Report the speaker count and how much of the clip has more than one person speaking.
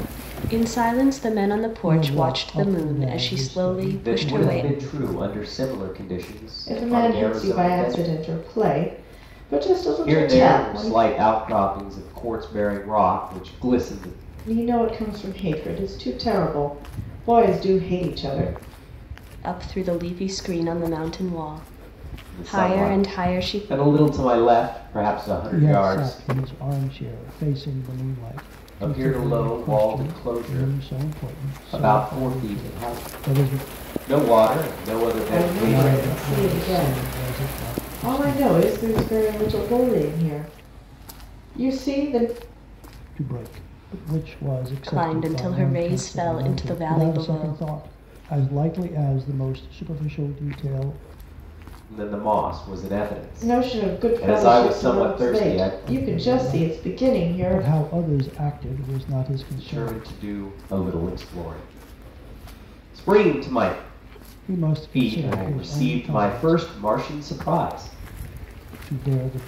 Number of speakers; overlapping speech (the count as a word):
four, about 34%